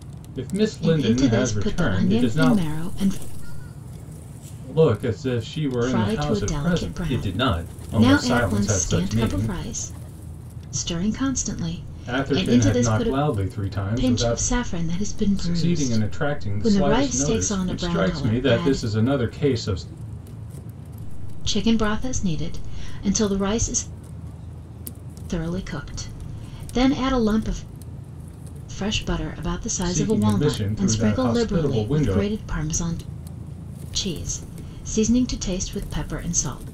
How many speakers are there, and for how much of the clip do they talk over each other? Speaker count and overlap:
three, about 42%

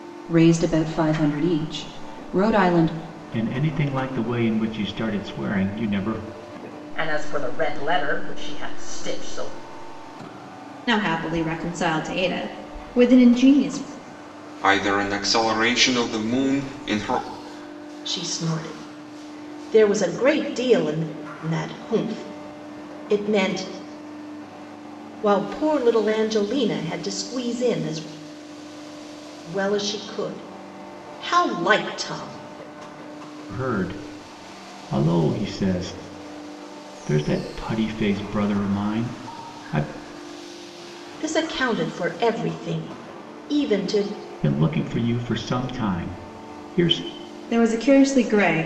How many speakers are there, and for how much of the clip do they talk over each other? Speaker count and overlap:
six, no overlap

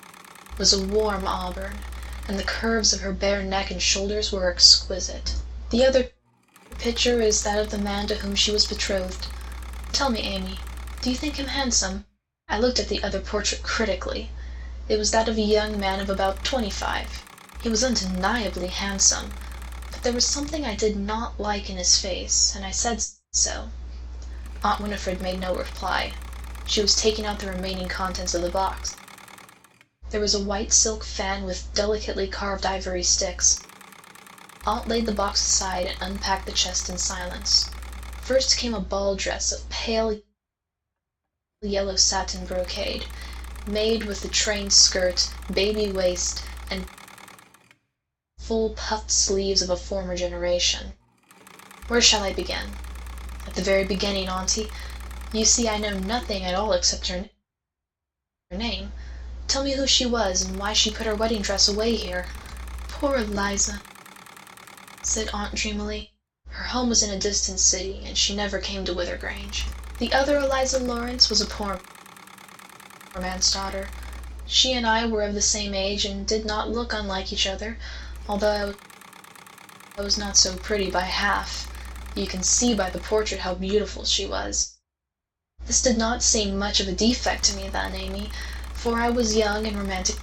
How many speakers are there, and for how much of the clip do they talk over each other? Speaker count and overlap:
one, no overlap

